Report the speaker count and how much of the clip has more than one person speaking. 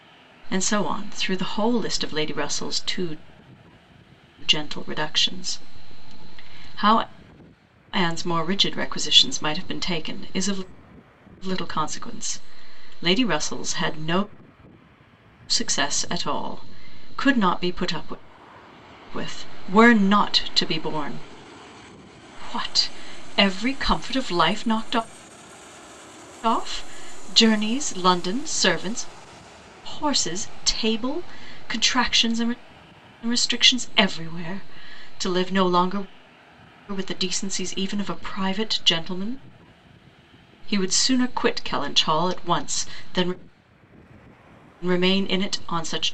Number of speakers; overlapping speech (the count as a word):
one, no overlap